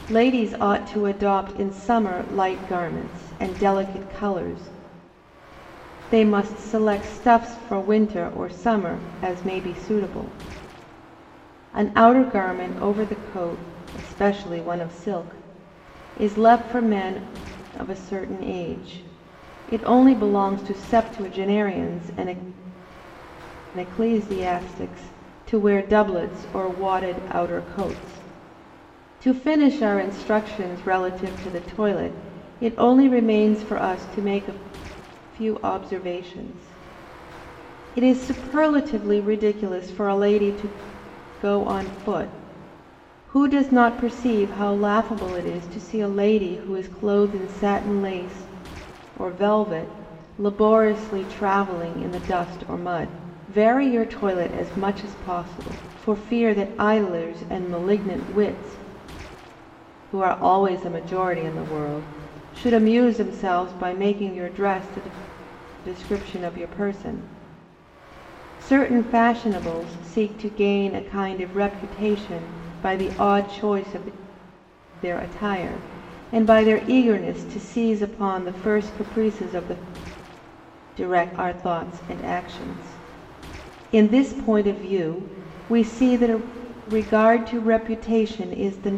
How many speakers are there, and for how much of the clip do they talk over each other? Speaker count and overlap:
1, no overlap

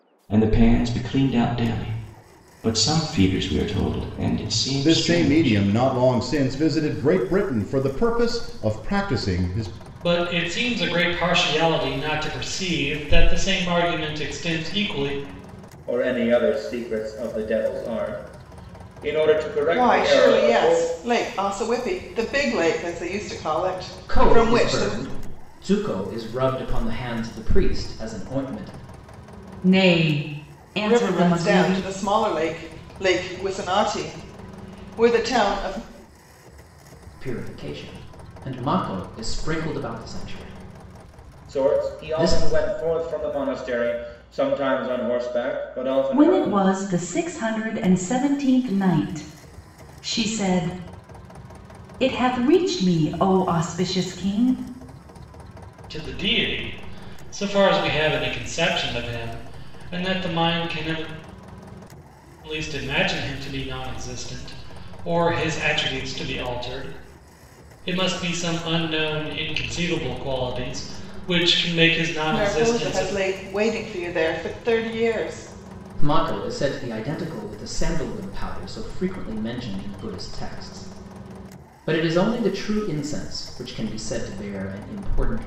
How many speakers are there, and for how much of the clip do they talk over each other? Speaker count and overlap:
7, about 7%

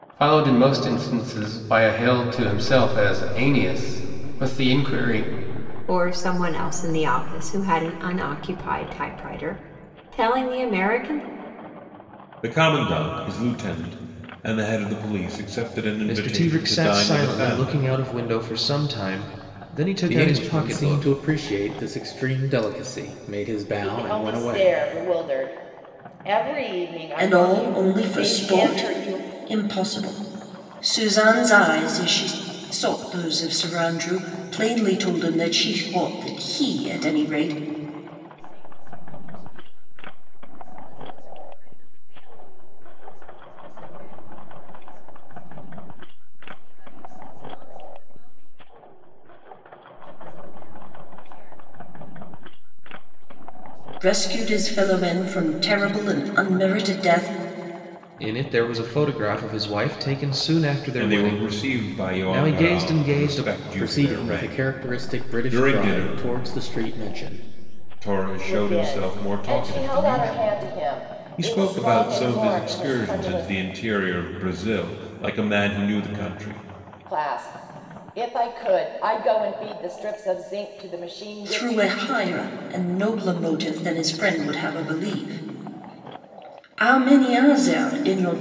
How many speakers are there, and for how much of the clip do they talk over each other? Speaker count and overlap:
8, about 27%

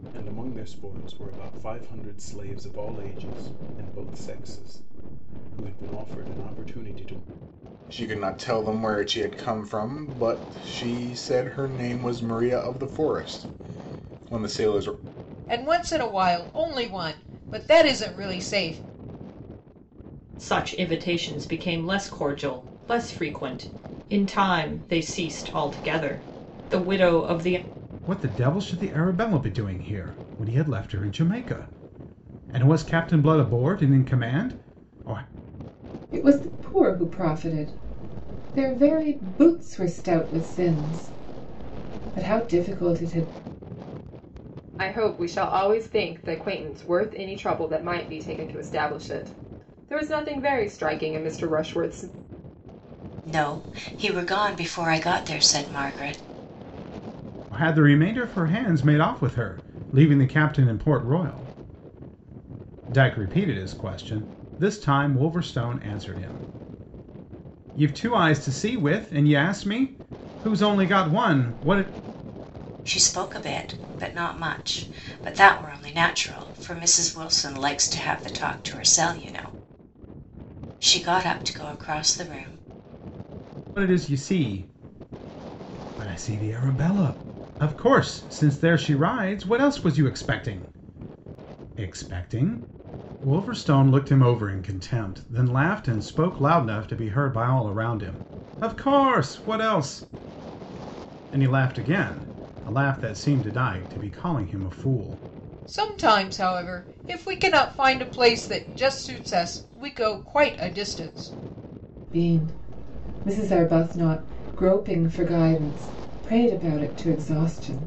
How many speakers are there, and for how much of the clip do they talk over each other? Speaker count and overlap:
8, no overlap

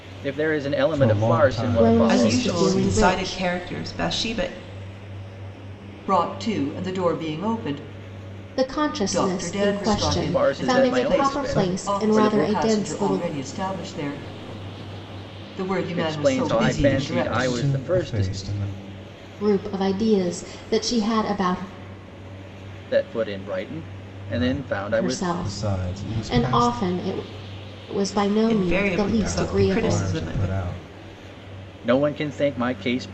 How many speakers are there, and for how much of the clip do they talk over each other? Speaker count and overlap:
5, about 41%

